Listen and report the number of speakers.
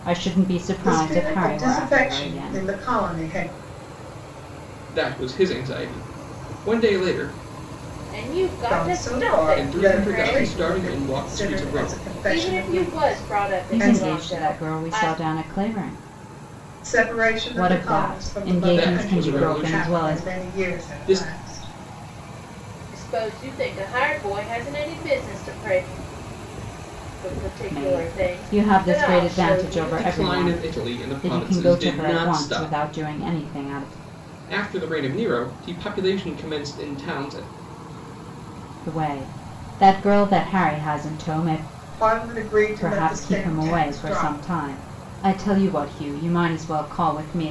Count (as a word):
four